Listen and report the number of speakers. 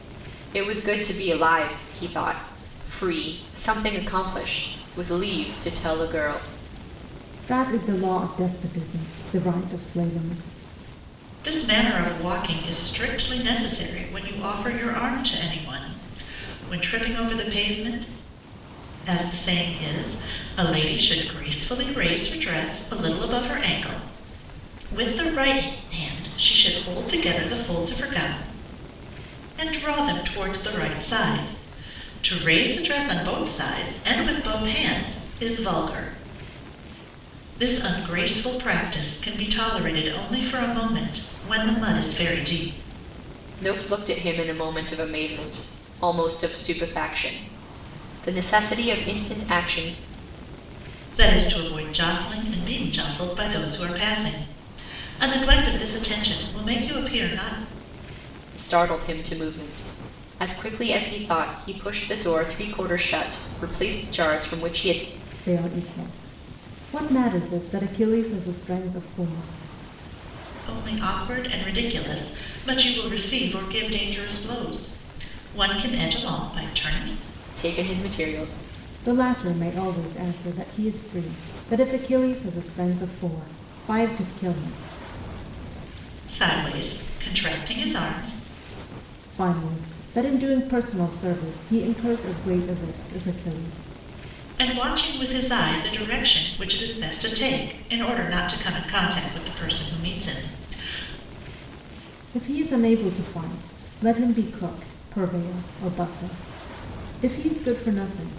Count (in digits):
3